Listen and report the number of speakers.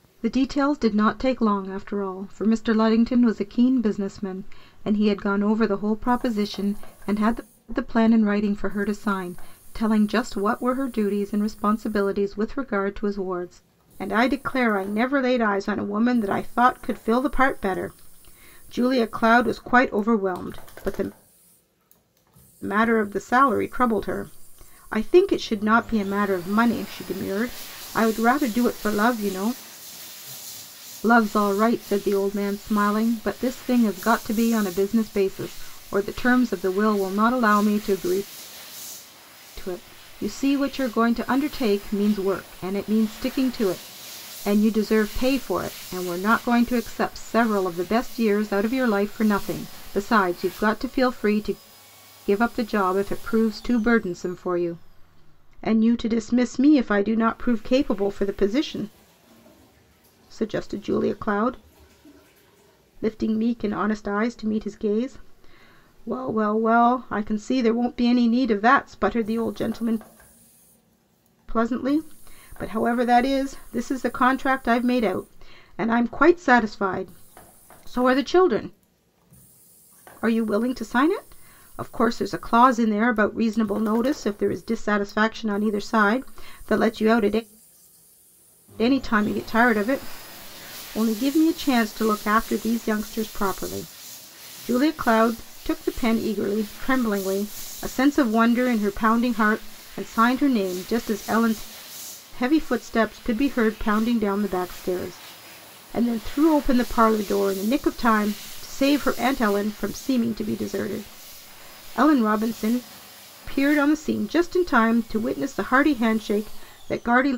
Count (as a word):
one